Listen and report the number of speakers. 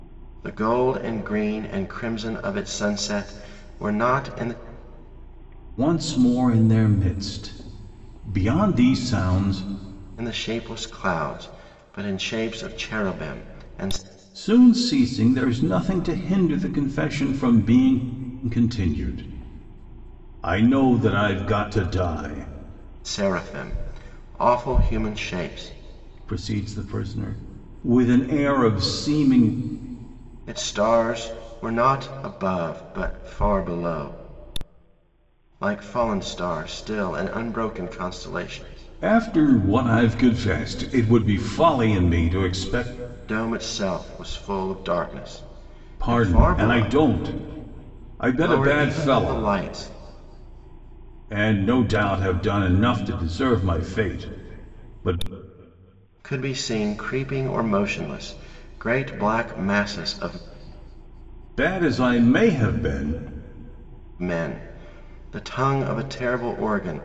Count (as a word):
two